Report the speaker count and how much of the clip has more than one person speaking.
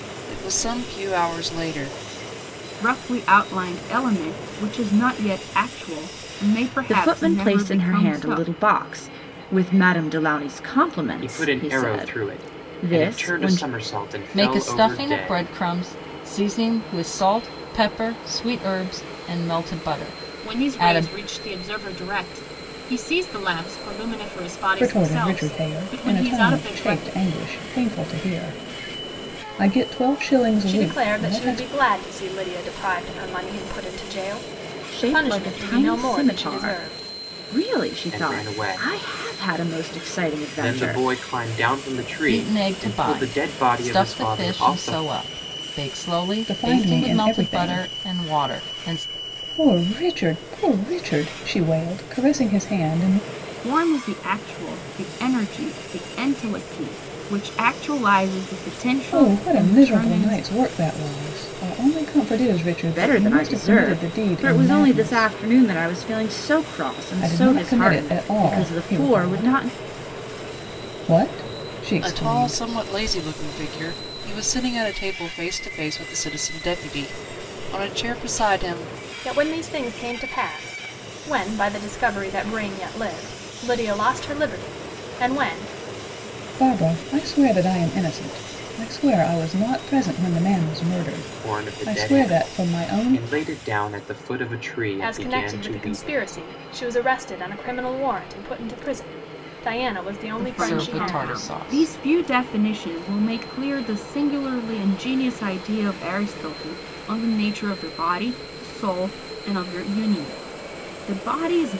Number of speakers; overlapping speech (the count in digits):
8, about 29%